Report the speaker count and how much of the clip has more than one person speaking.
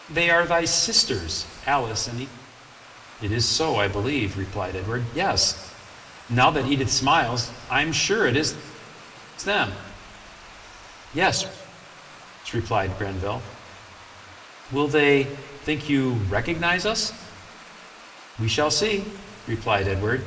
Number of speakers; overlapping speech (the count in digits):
1, no overlap